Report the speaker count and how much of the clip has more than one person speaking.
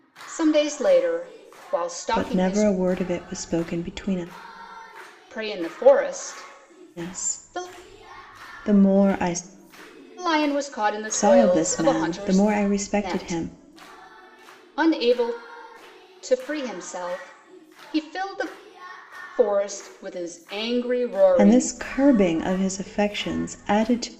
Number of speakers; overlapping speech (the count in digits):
2, about 15%